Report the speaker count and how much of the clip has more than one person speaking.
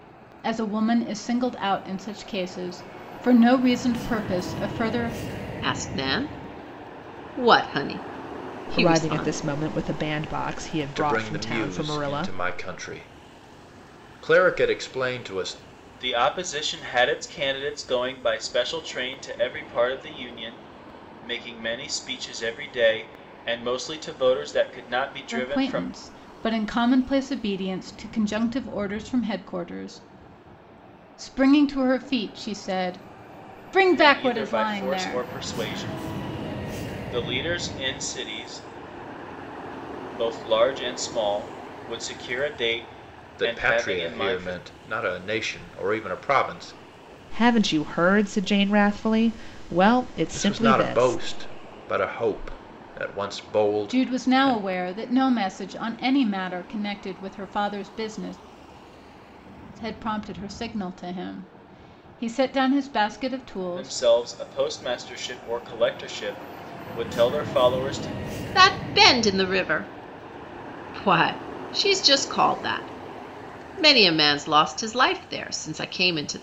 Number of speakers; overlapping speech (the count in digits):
5, about 10%